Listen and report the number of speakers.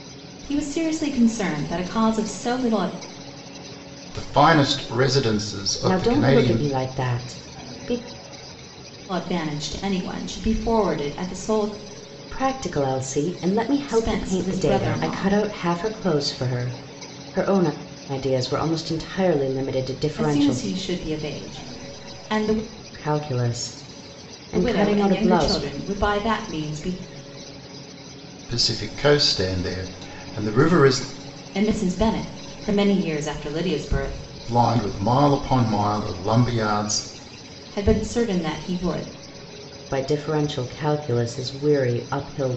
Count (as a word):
three